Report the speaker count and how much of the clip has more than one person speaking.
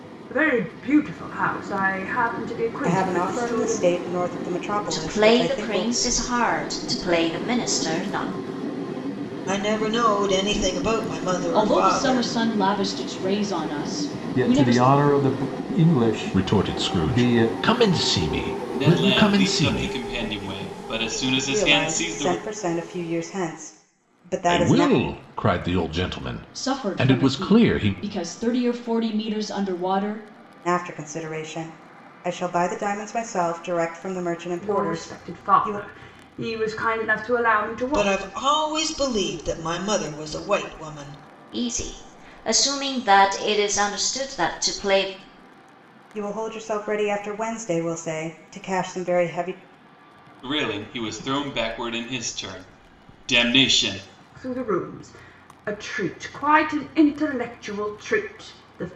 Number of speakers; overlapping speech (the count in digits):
8, about 18%